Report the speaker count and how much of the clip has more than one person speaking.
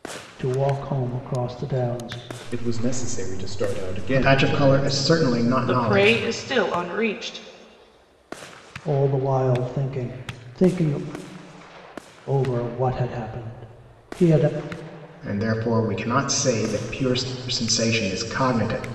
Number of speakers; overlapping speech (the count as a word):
four, about 8%